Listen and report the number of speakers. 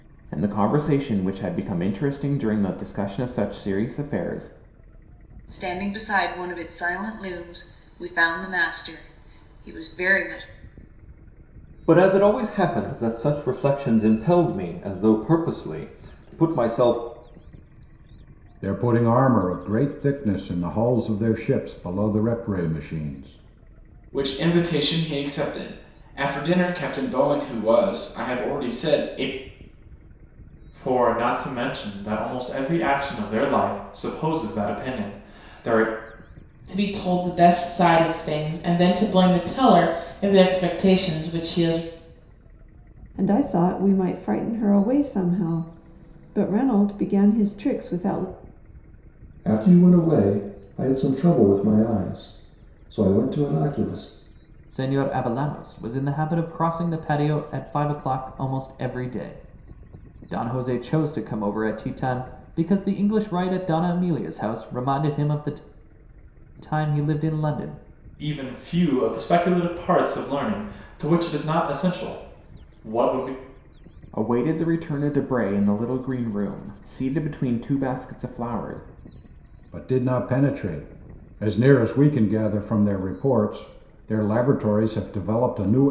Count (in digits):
10